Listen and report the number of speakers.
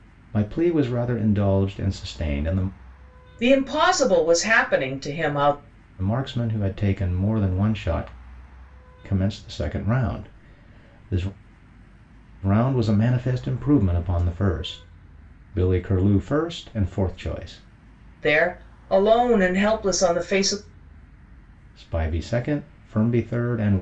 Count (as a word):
two